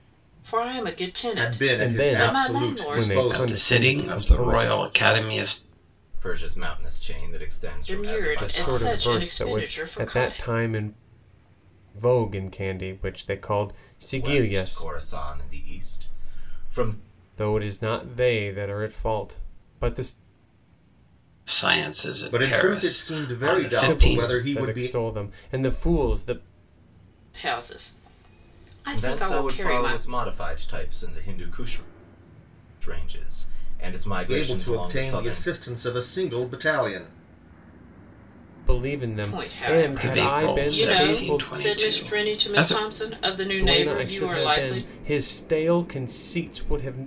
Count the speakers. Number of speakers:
five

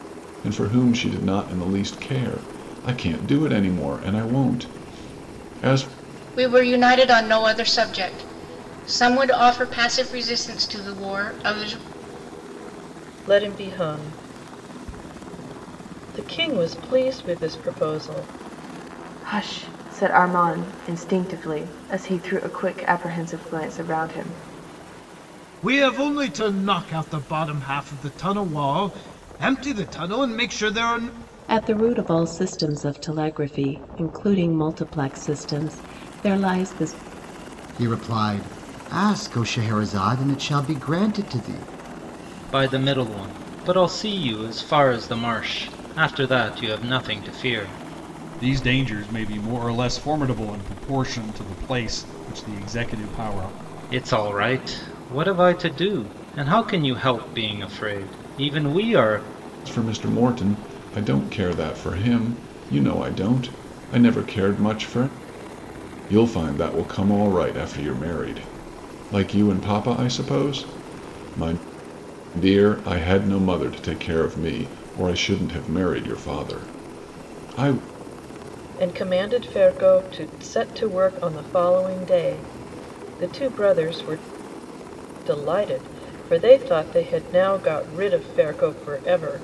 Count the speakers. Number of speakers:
nine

